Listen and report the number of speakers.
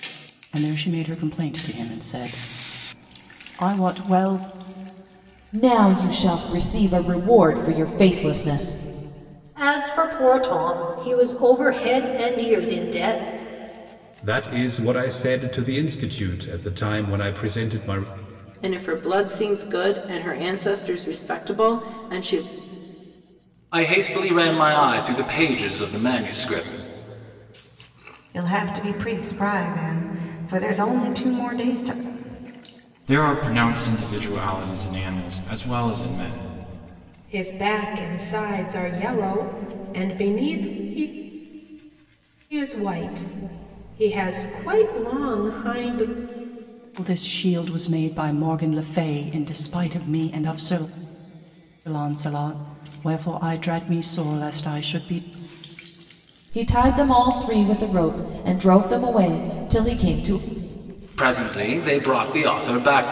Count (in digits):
9